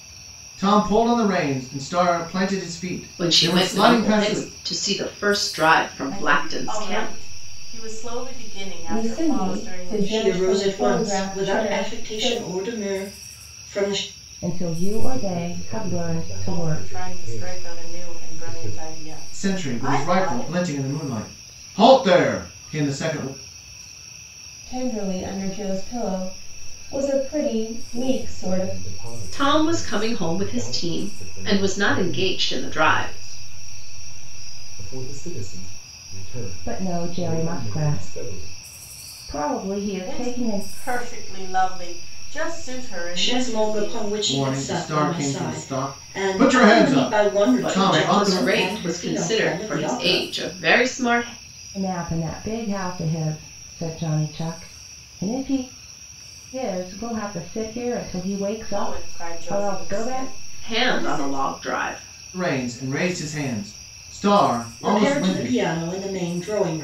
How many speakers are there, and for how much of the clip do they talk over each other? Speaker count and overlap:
seven, about 43%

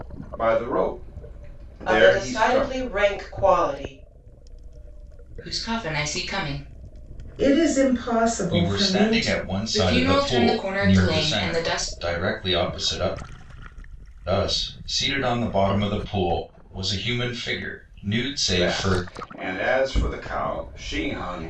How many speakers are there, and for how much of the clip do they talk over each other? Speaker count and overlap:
five, about 22%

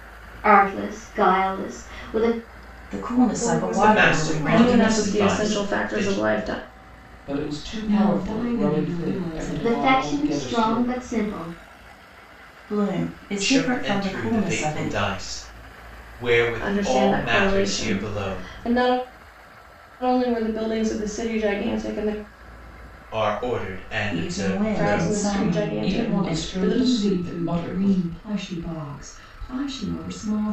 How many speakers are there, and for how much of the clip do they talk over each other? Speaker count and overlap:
seven, about 44%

